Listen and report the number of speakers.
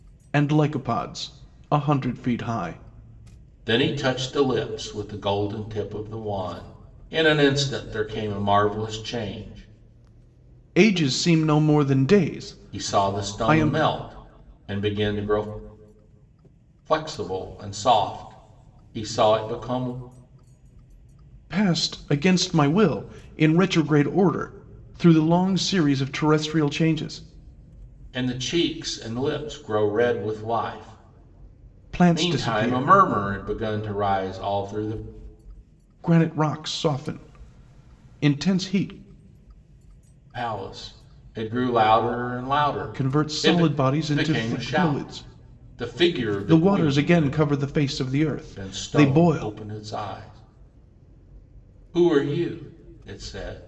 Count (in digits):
2